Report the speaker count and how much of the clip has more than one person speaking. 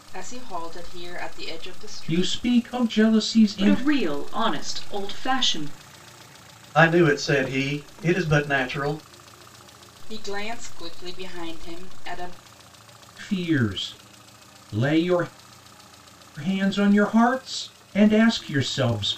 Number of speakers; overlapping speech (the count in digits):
4, about 4%